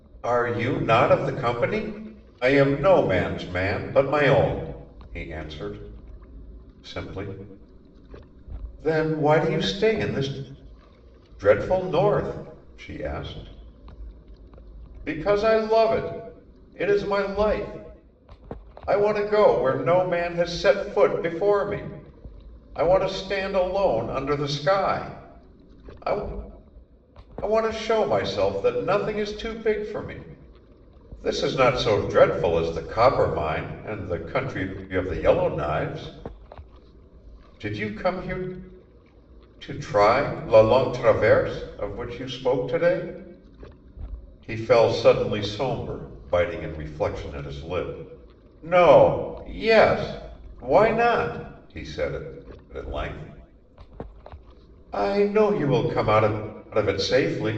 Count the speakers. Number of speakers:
1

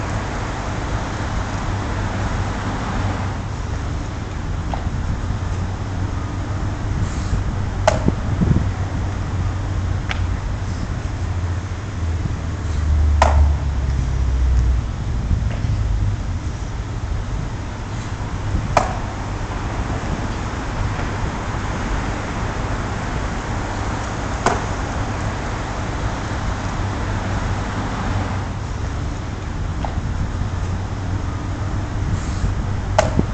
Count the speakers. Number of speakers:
0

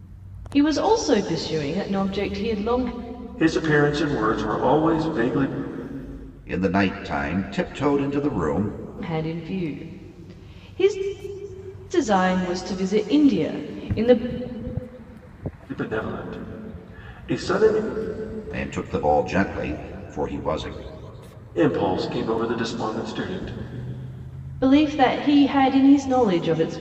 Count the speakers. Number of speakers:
3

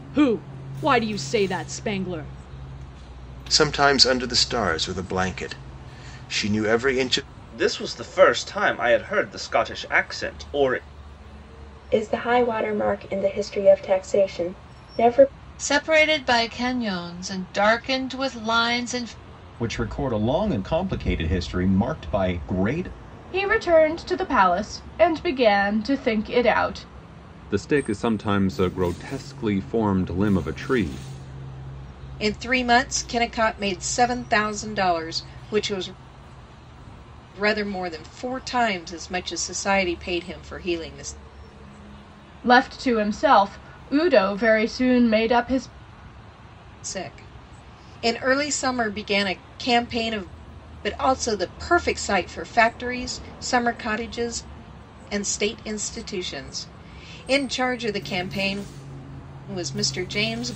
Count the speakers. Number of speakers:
9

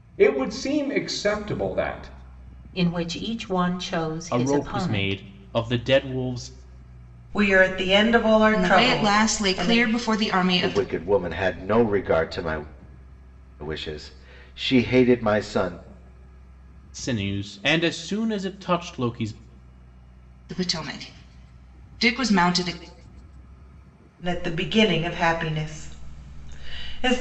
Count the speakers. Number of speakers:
6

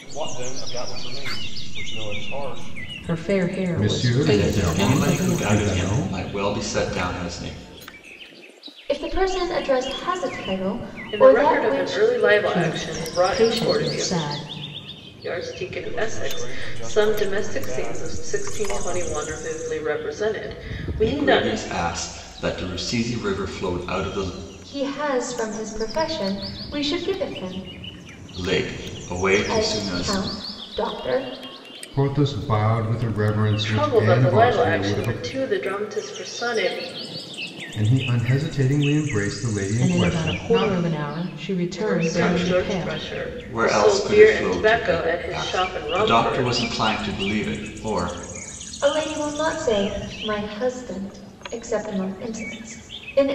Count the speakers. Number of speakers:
6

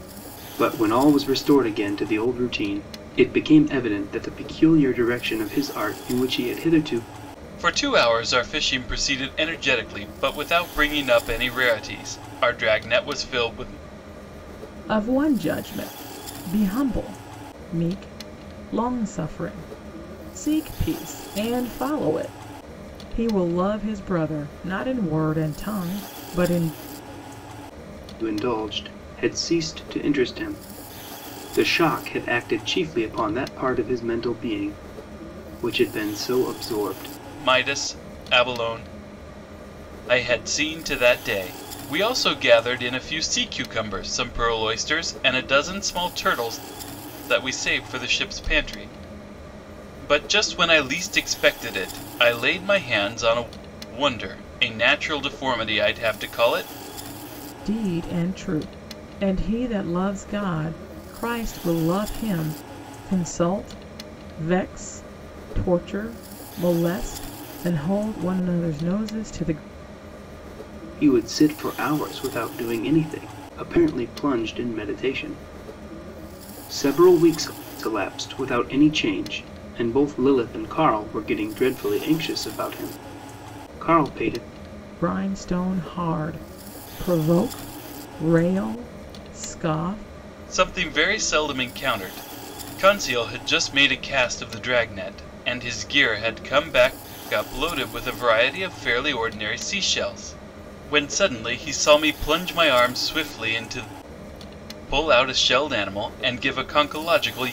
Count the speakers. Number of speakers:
3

